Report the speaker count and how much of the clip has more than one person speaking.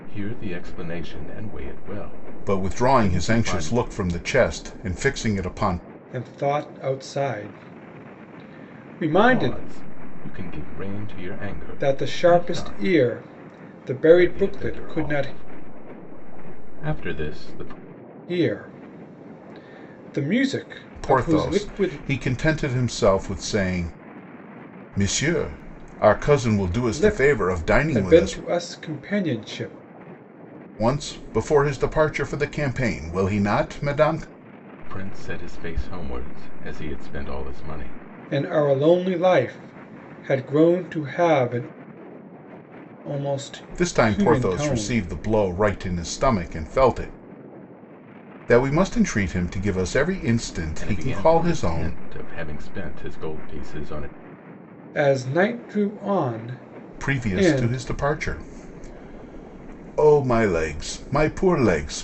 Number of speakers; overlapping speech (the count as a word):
three, about 17%